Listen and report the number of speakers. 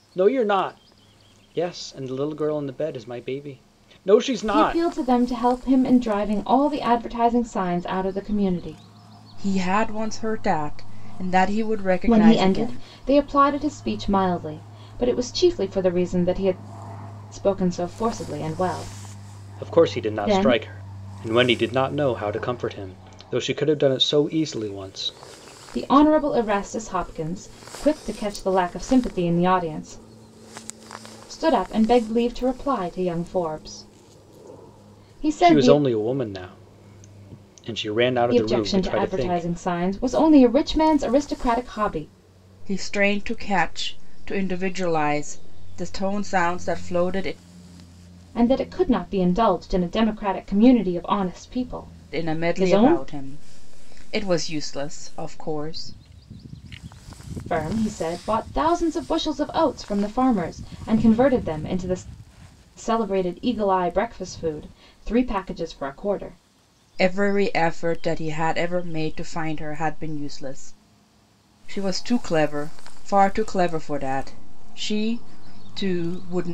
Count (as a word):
three